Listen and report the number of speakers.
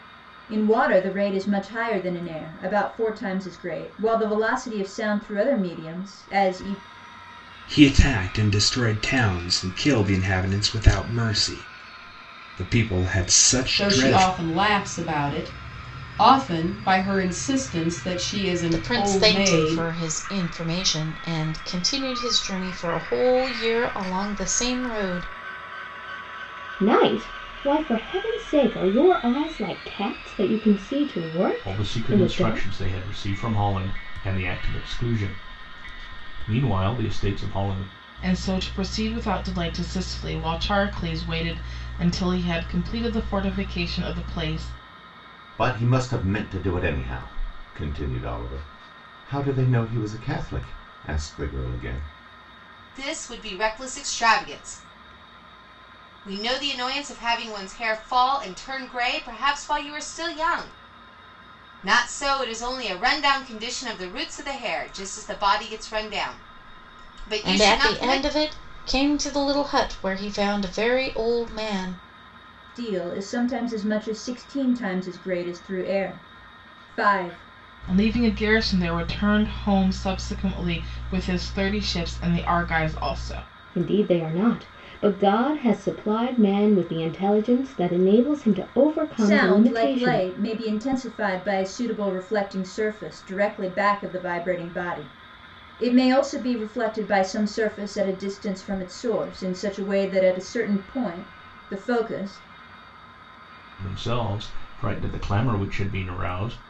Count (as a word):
nine